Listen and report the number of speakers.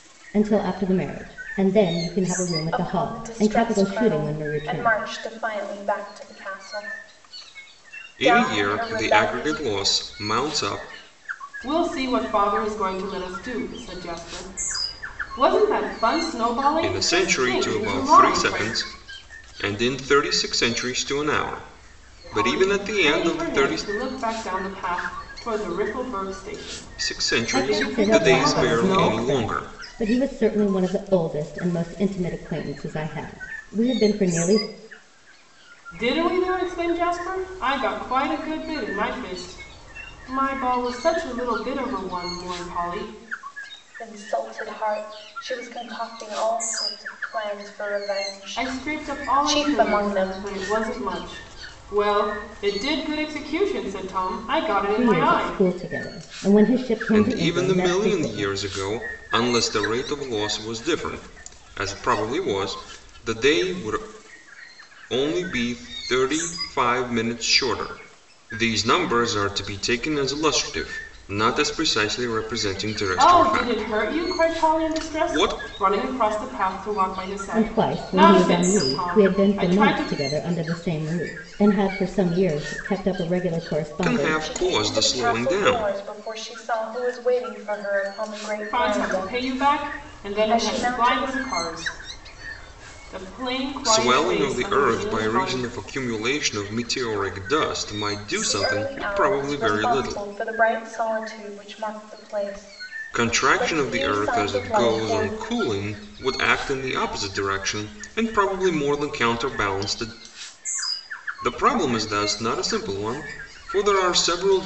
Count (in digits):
4